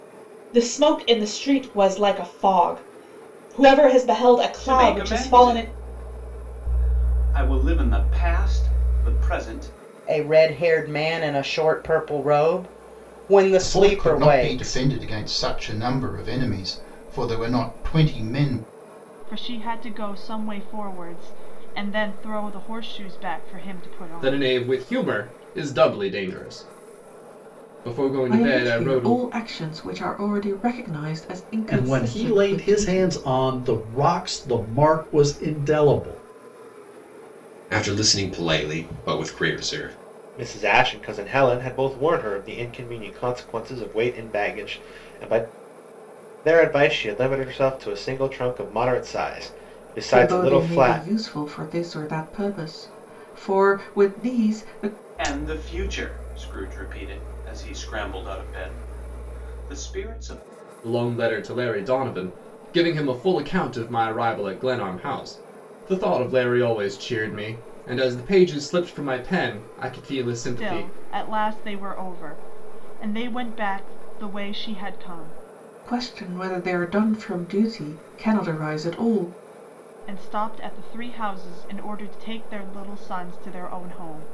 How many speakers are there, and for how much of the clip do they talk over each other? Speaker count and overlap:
10, about 8%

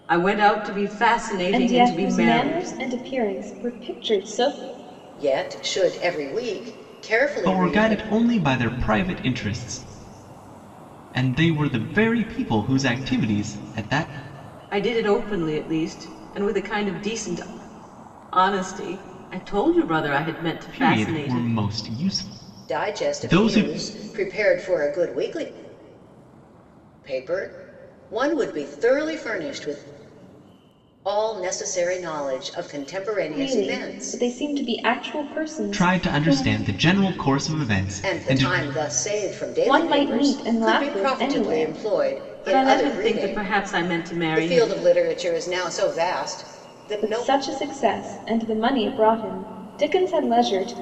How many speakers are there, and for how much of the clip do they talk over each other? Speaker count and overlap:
4, about 20%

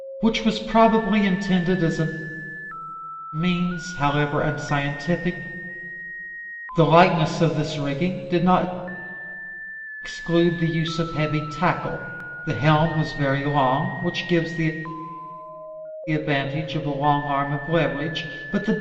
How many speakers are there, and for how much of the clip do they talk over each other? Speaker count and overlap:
1, no overlap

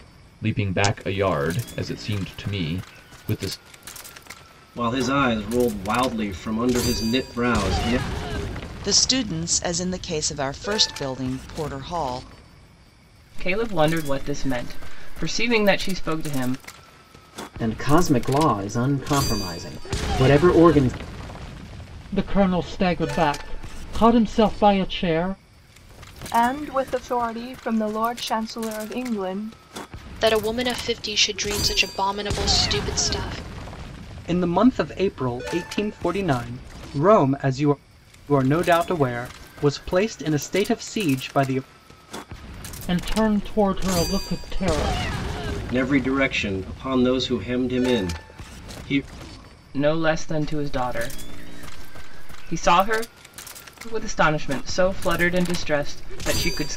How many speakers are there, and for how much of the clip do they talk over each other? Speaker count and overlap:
9, no overlap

